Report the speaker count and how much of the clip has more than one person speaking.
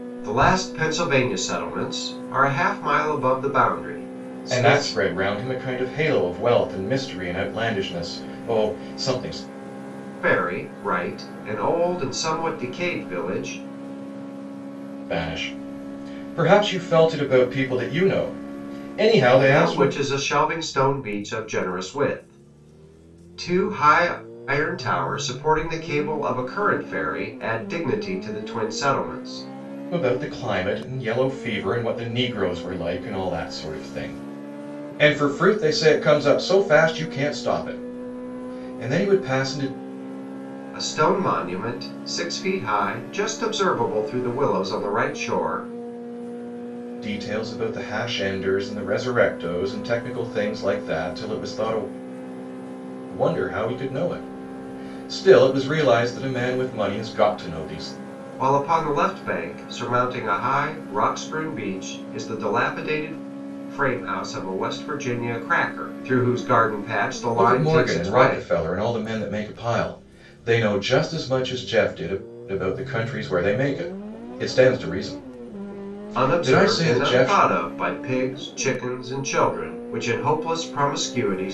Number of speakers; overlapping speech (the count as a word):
two, about 4%